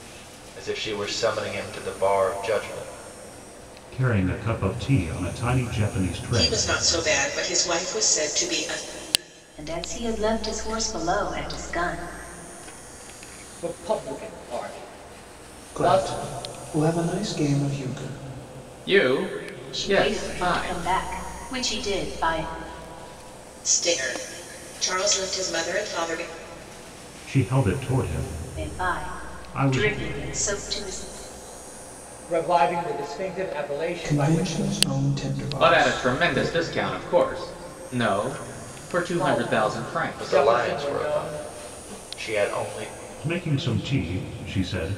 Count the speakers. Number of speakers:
seven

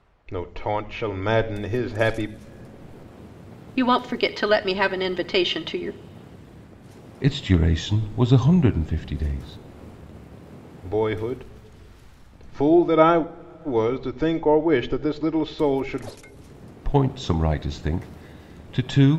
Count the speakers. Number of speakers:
three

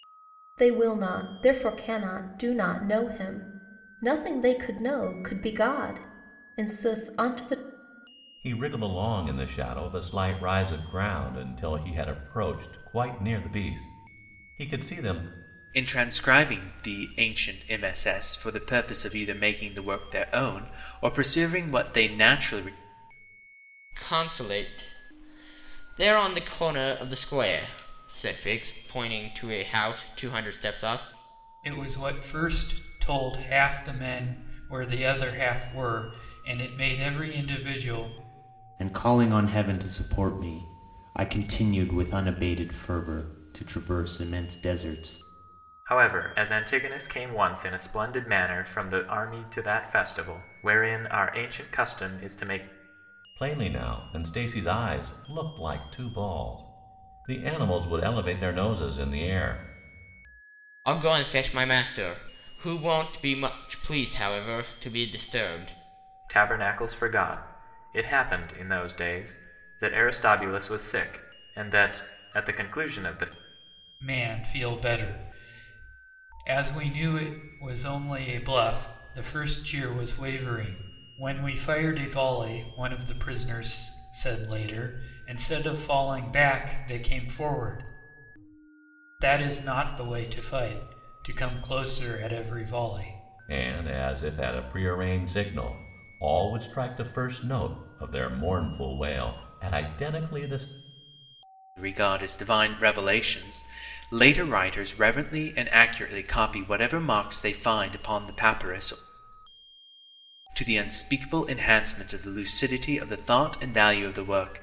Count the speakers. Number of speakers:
seven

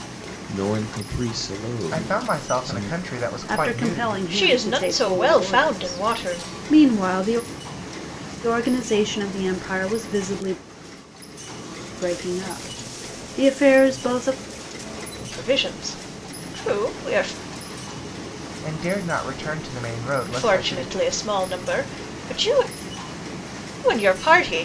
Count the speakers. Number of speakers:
four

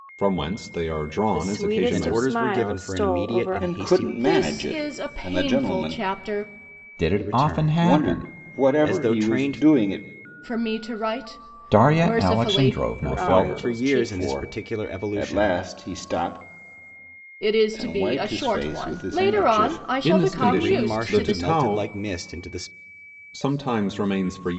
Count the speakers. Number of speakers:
six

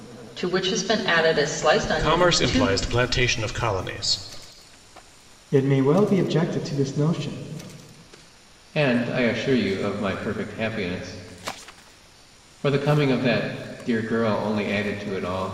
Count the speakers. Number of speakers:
four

